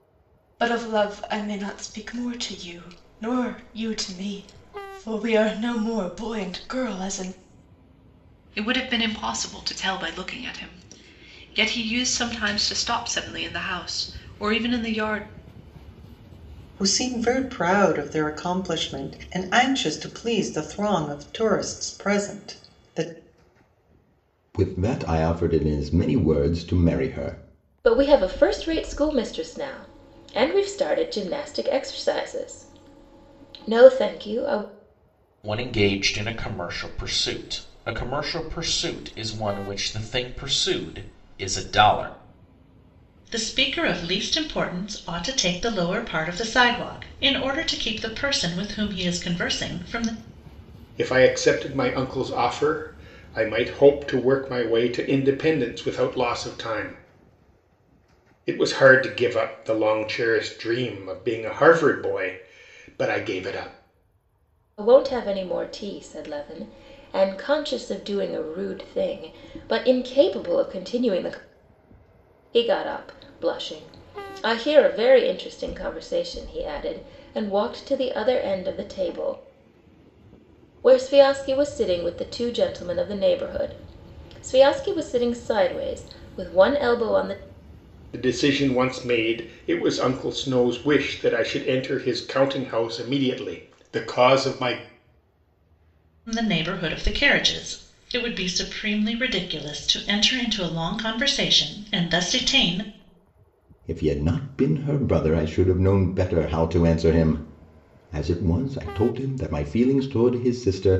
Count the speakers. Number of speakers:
eight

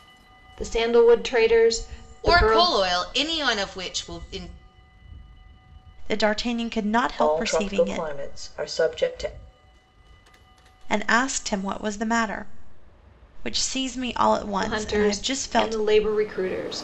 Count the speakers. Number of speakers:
four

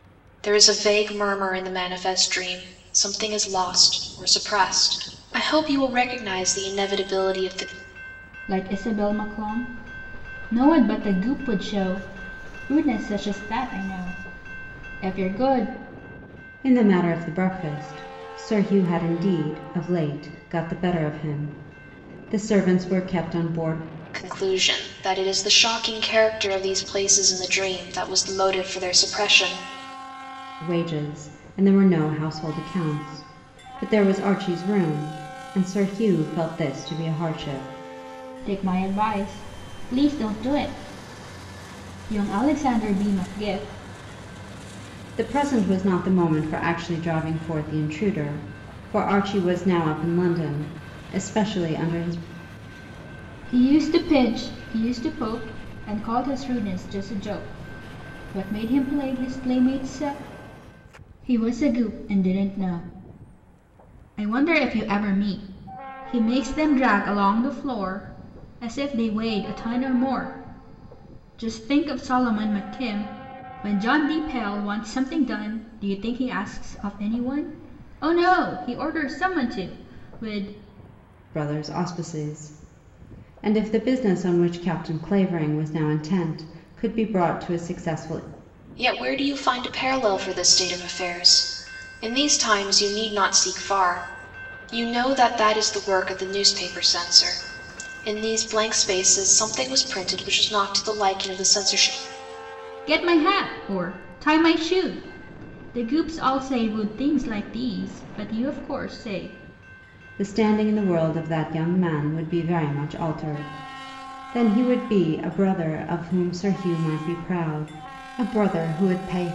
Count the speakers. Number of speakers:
three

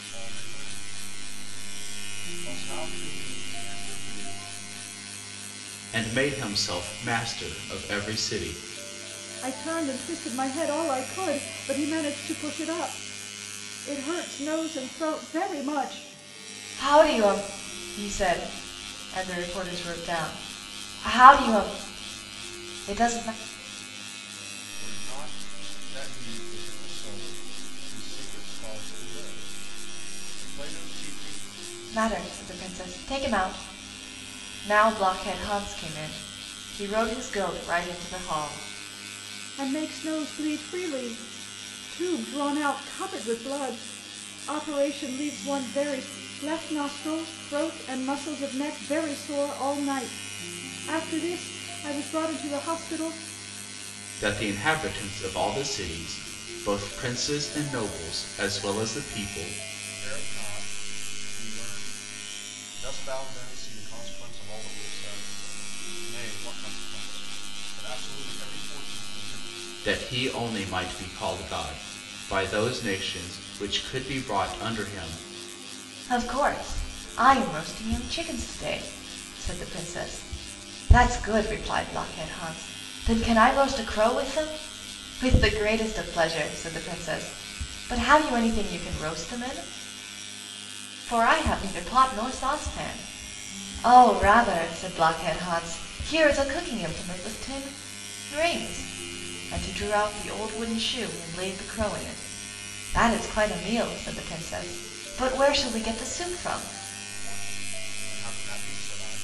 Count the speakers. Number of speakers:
four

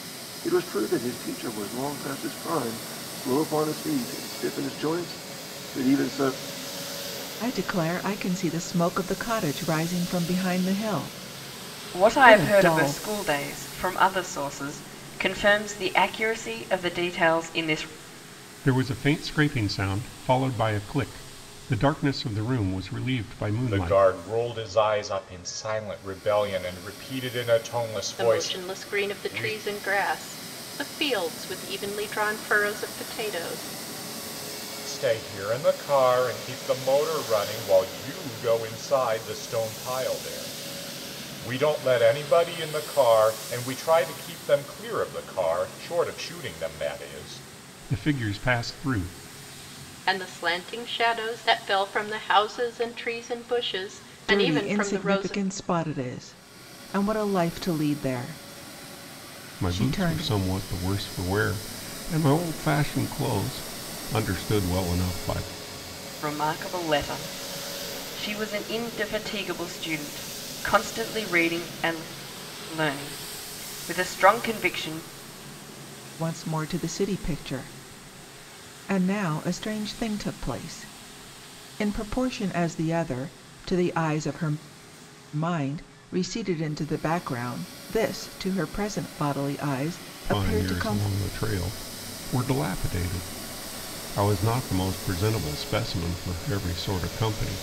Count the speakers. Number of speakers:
six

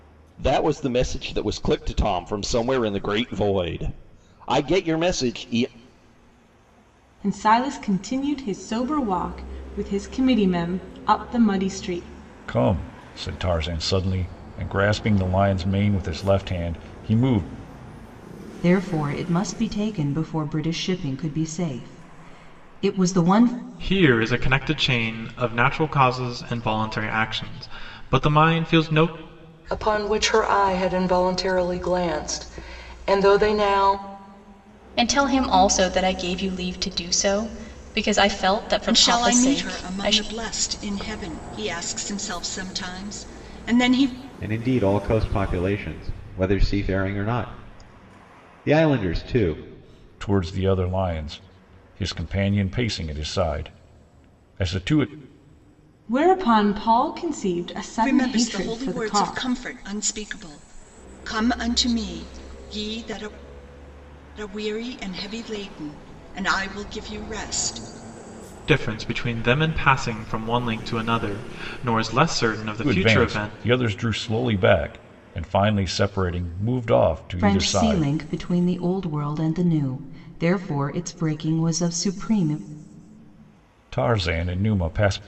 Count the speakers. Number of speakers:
nine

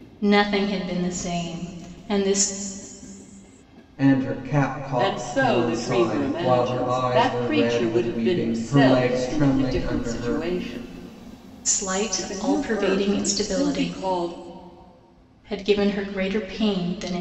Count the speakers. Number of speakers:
three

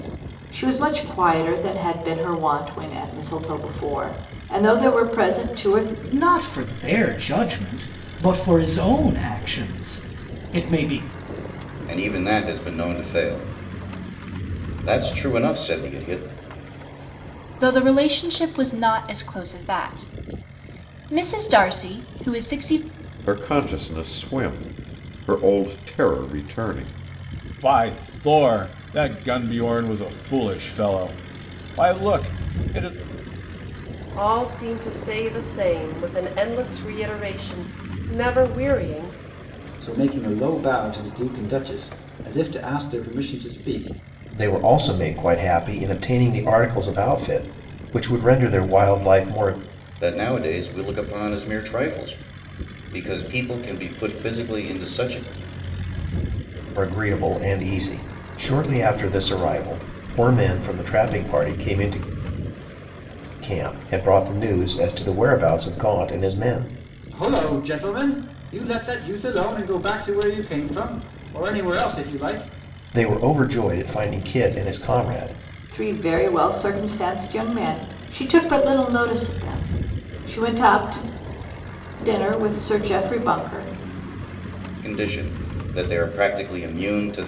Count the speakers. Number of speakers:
nine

